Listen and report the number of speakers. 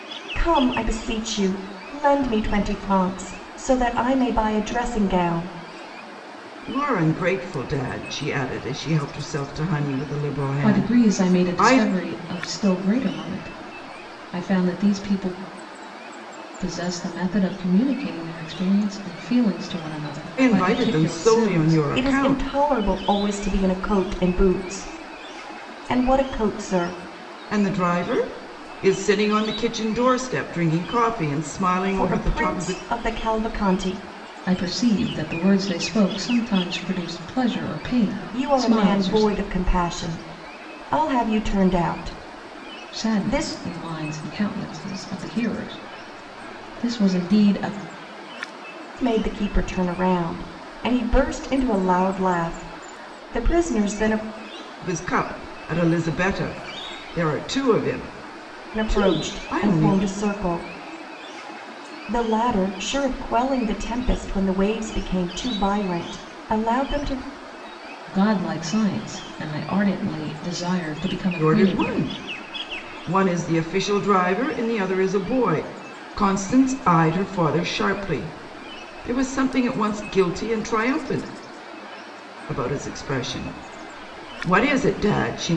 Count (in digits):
3